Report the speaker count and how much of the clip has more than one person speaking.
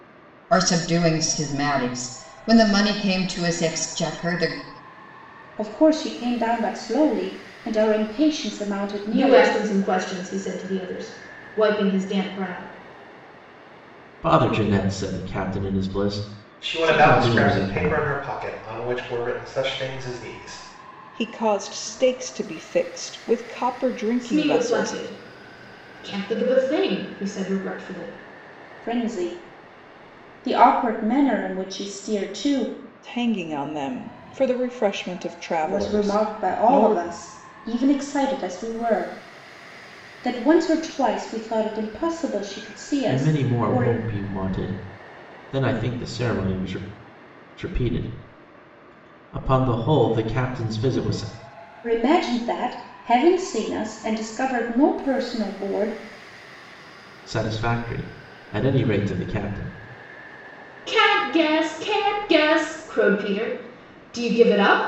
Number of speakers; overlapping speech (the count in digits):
6, about 8%